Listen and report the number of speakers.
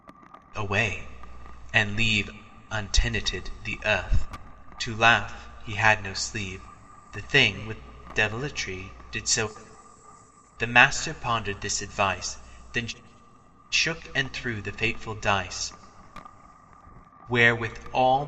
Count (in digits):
1